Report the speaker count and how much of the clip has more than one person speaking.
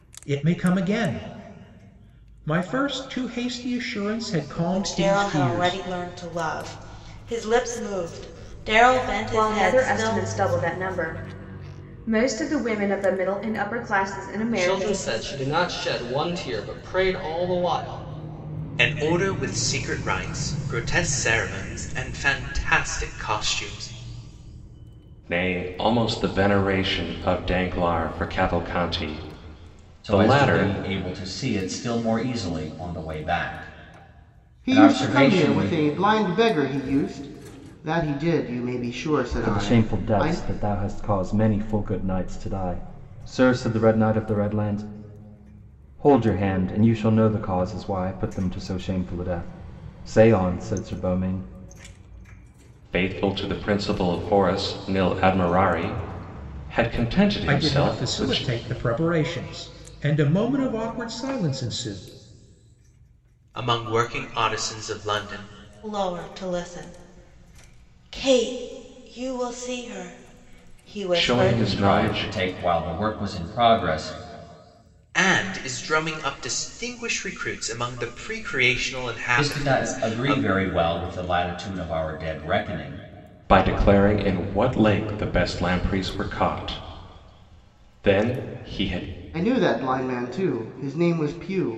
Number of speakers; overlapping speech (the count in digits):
9, about 10%